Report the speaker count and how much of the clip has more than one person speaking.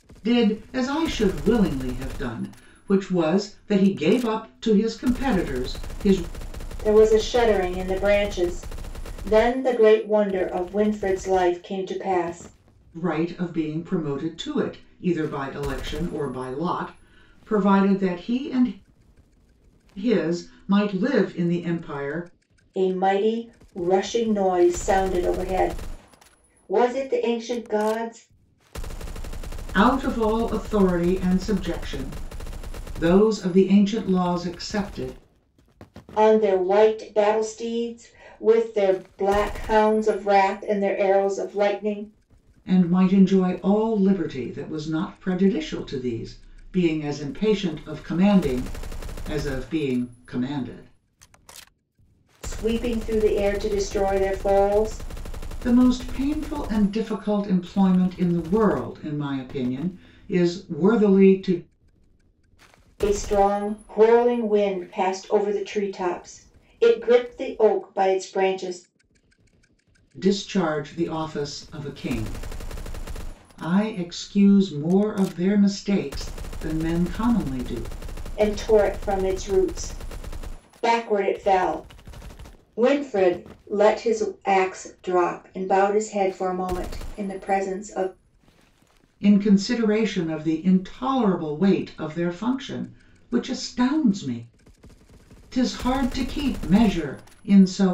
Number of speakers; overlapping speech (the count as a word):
two, no overlap